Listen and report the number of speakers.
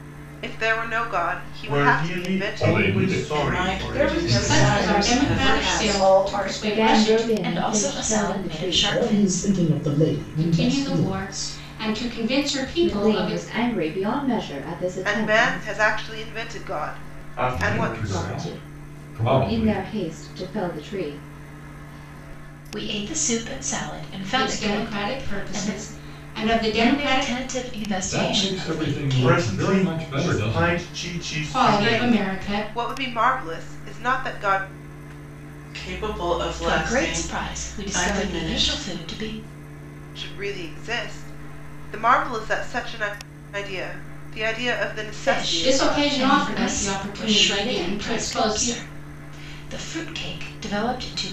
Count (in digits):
9